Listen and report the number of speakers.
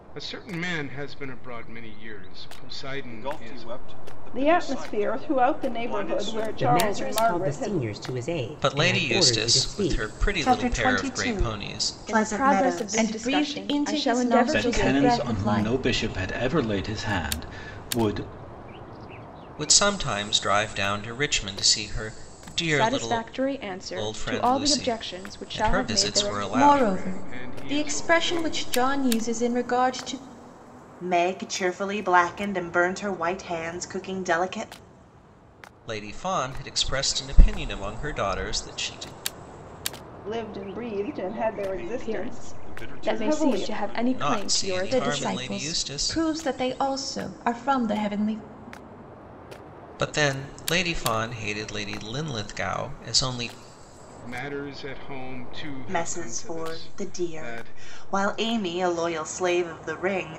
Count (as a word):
nine